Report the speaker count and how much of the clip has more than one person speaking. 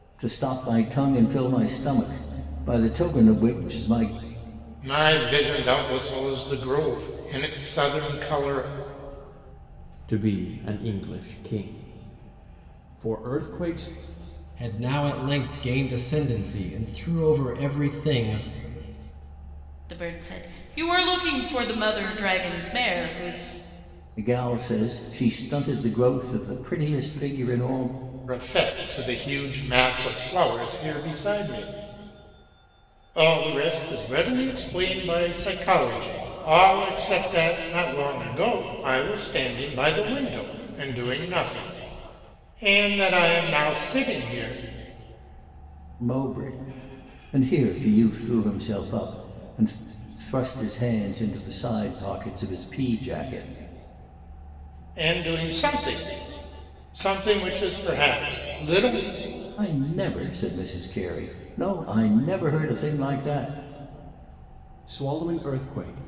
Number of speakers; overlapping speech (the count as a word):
five, no overlap